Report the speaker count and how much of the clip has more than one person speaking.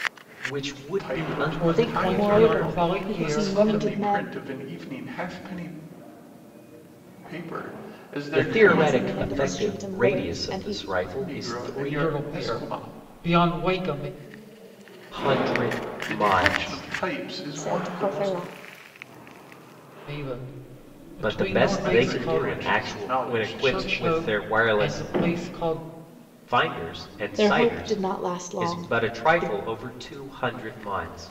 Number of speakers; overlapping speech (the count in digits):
4, about 50%